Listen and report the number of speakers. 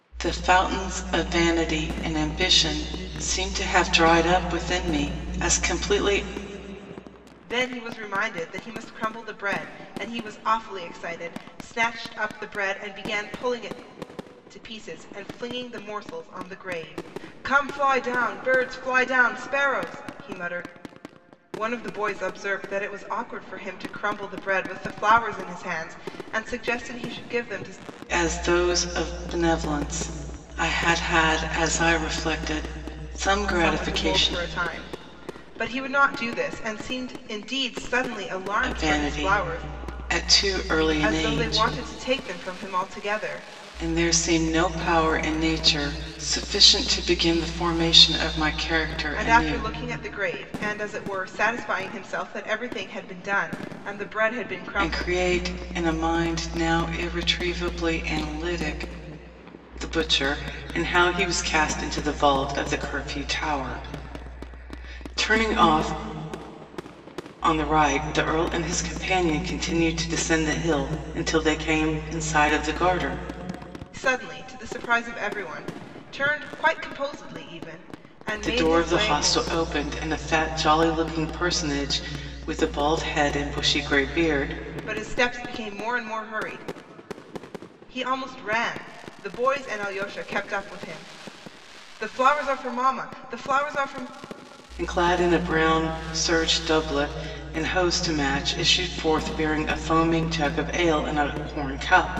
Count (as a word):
two